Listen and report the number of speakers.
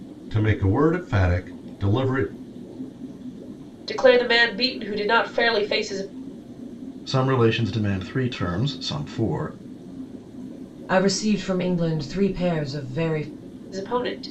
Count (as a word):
four